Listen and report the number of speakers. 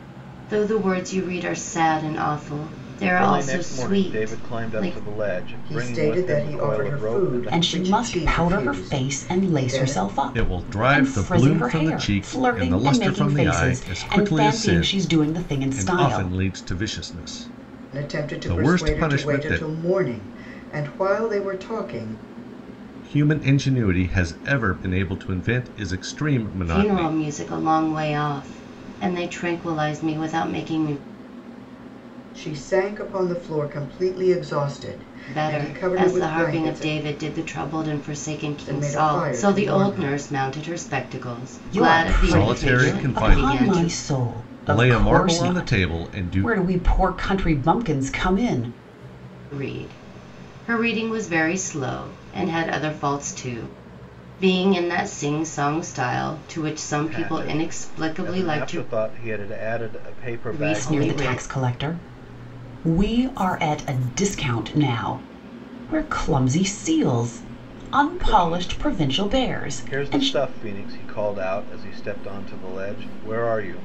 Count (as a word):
five